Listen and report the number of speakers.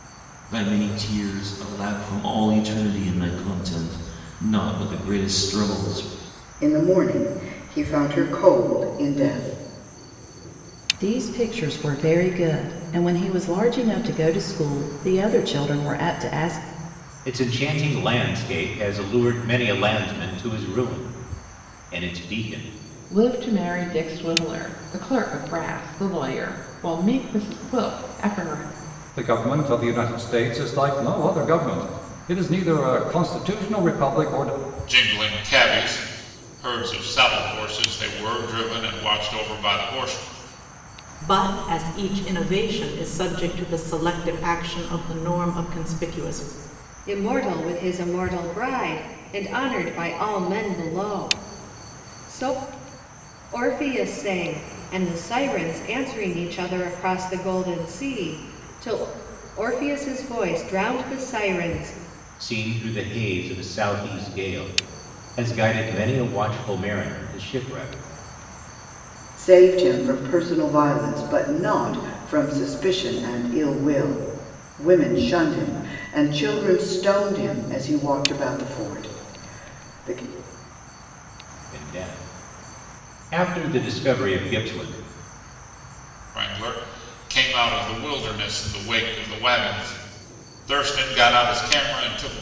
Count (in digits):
9